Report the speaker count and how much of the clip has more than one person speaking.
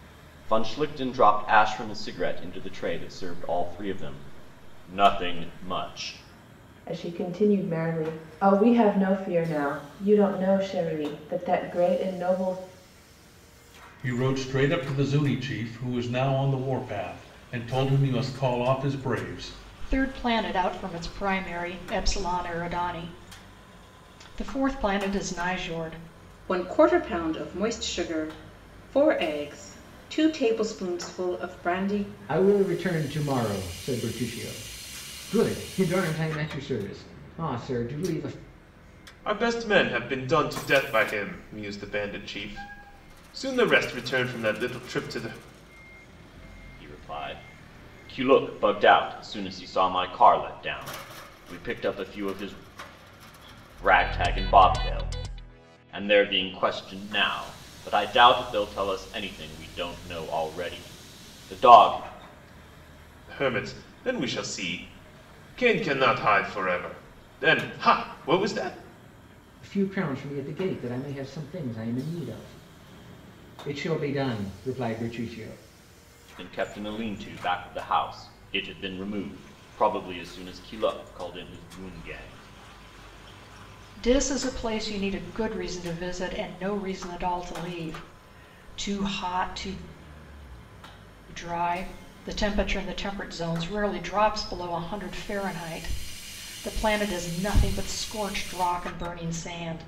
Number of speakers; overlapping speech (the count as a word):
seven, no overlap